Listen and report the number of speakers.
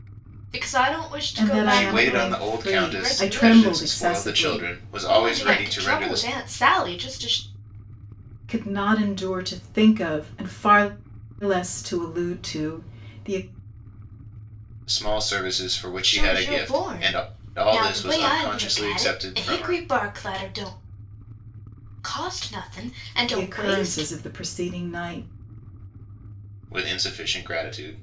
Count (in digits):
3